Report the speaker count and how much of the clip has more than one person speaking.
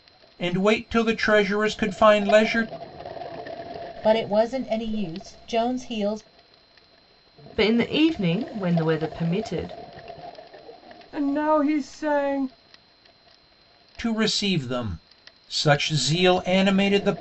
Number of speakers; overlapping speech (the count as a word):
four, no overlap